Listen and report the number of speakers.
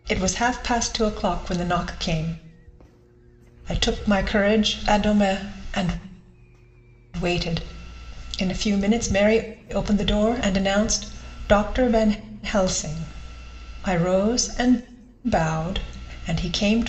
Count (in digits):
1